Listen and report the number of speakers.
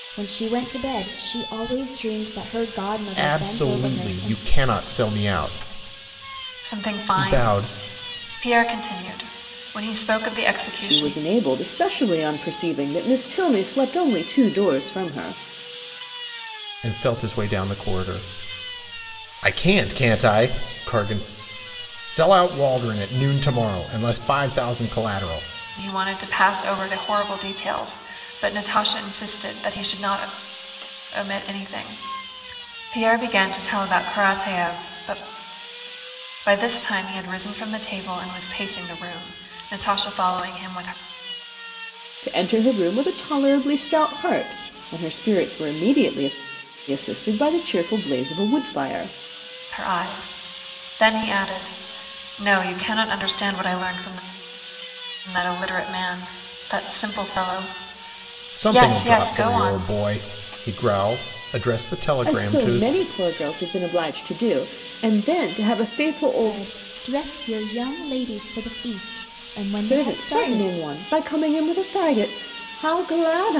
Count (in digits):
4